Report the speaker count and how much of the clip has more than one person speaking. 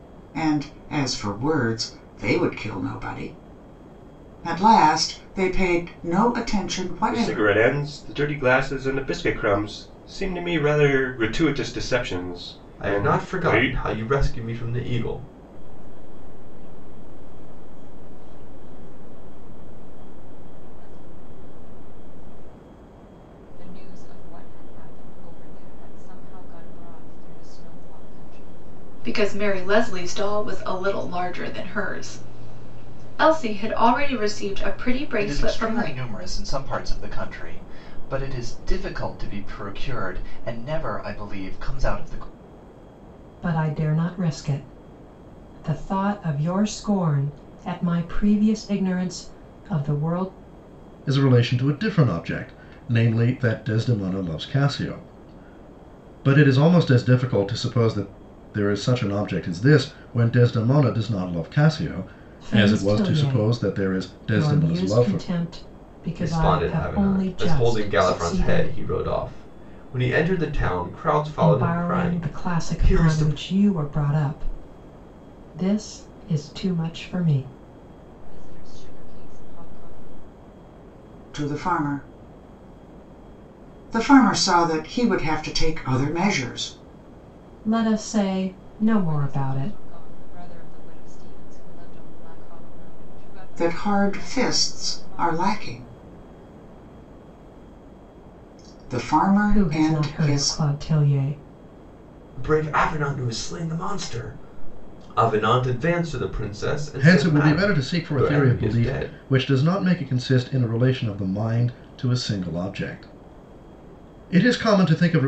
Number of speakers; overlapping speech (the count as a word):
nine, about 16%